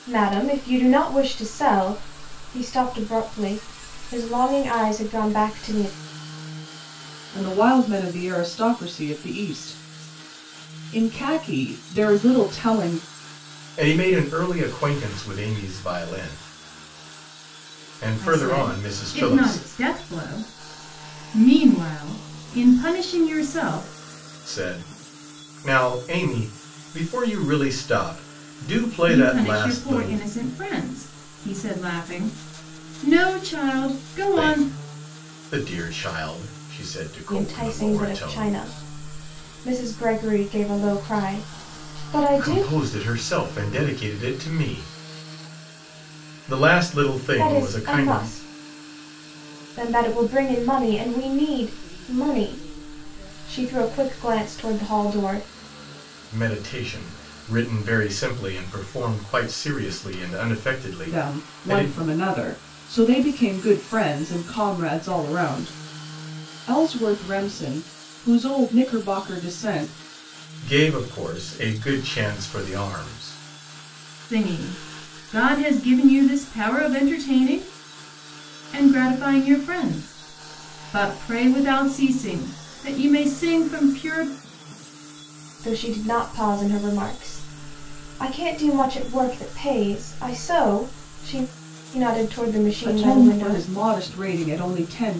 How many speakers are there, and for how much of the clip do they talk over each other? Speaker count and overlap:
4, about 8%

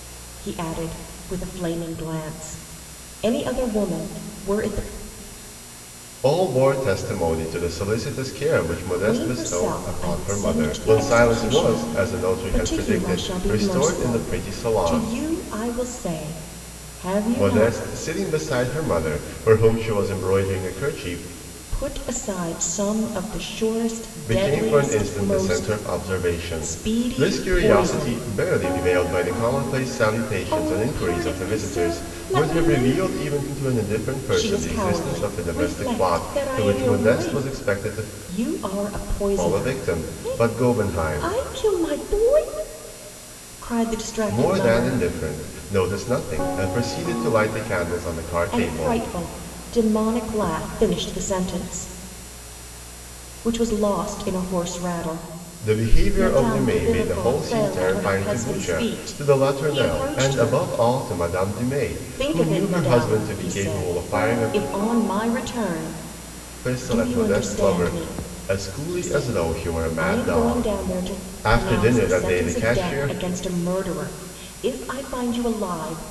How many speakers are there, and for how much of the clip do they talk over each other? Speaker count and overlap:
2, about 48%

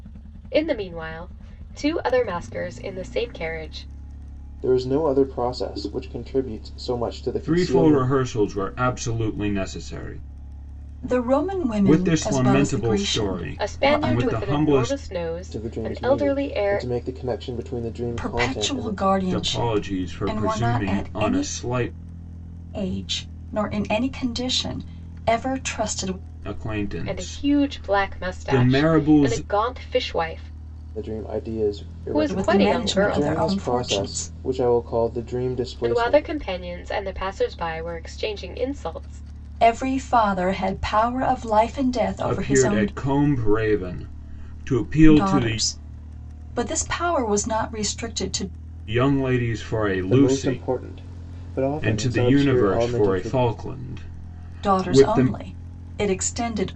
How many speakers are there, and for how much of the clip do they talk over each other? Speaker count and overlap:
4, about 31%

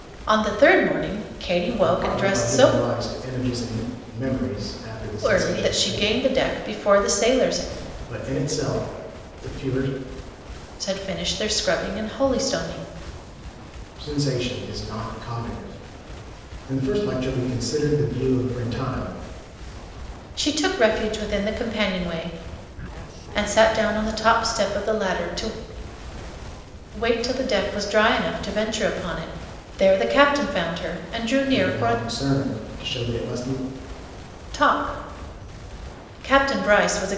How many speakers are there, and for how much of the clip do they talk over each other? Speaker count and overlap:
2, about 7%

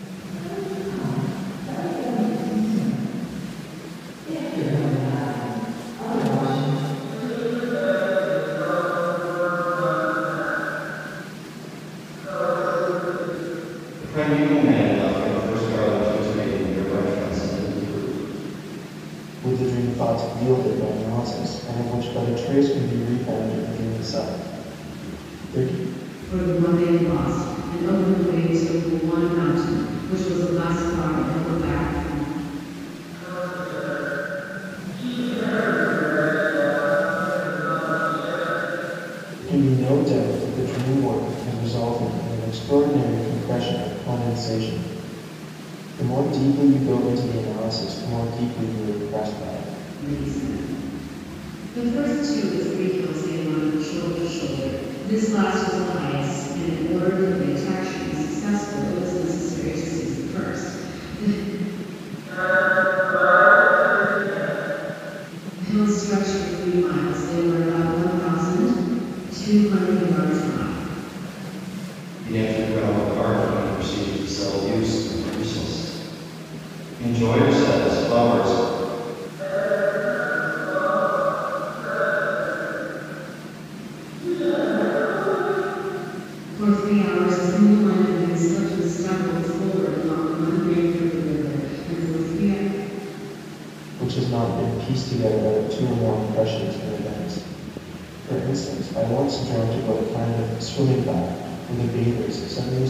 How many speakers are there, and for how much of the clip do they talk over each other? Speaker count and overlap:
5, no overlap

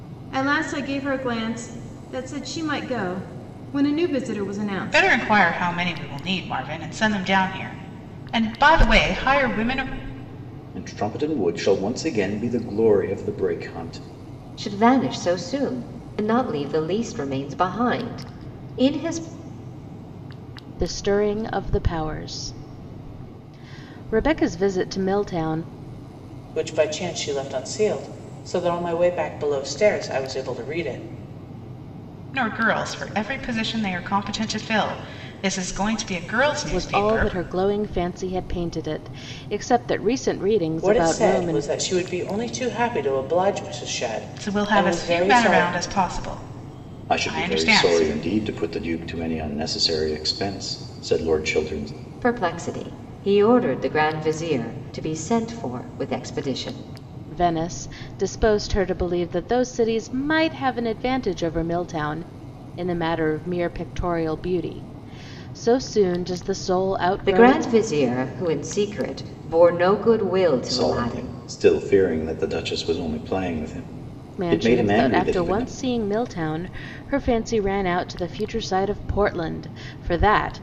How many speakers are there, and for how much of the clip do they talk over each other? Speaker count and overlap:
6, about 9%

